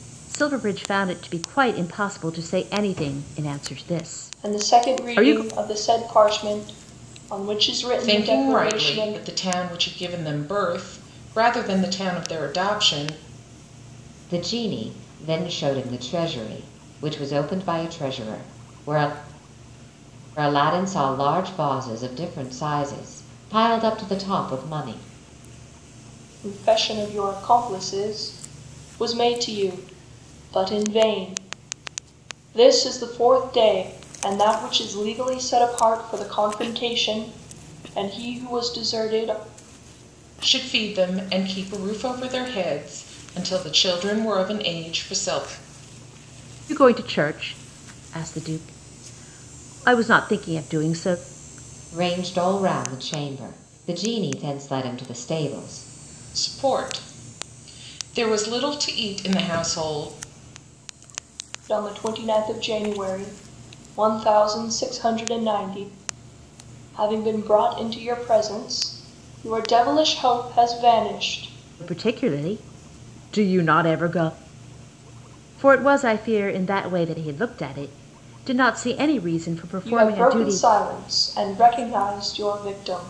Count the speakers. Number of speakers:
4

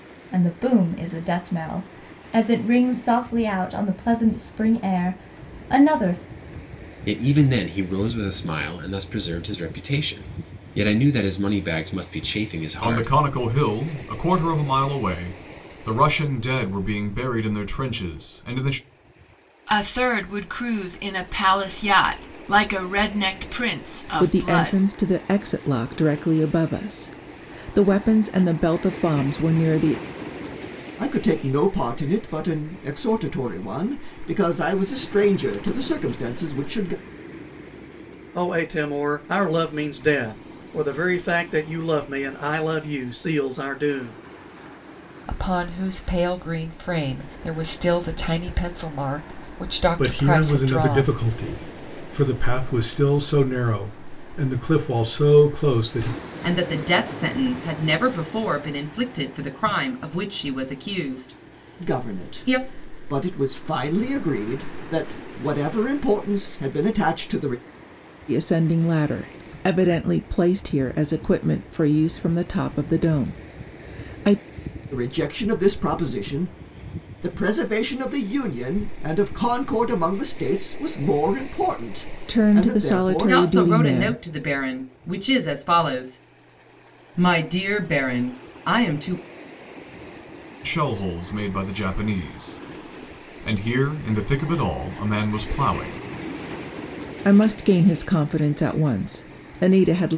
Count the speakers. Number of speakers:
10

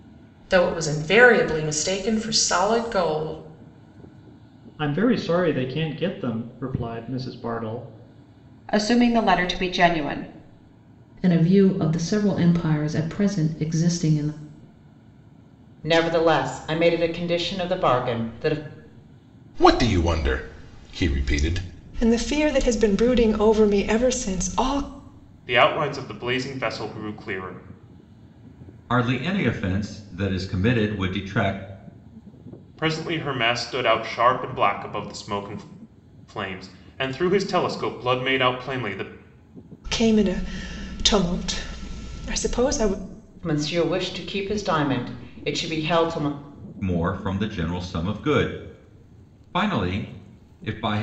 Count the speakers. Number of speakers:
9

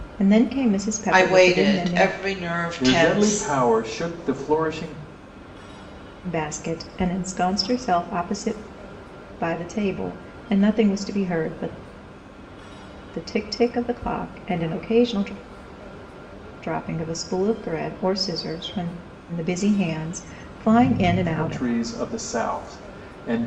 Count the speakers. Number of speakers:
3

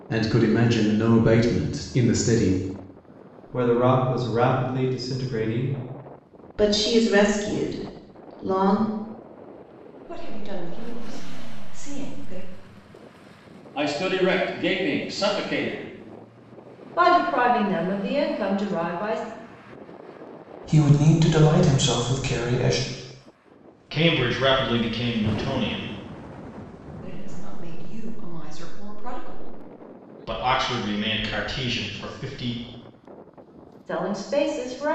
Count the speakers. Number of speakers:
8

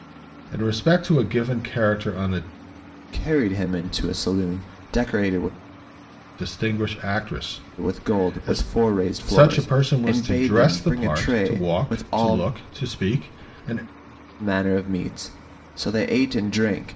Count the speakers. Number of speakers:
2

